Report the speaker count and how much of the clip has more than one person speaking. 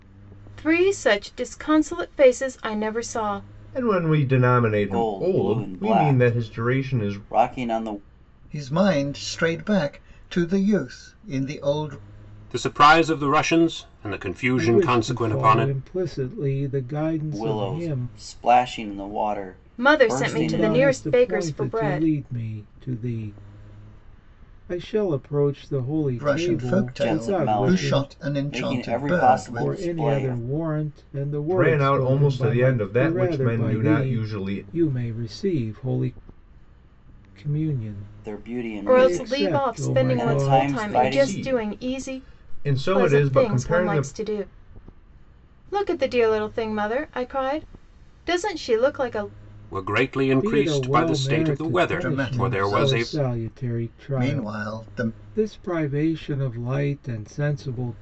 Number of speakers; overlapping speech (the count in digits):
6, about 42%